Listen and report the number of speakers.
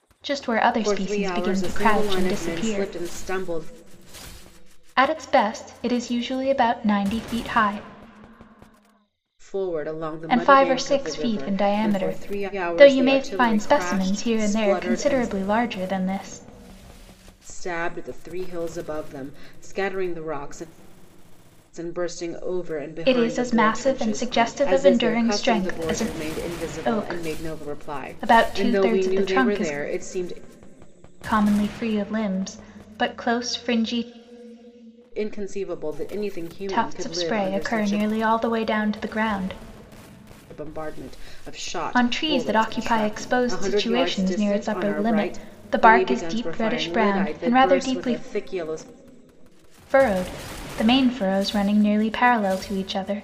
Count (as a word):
two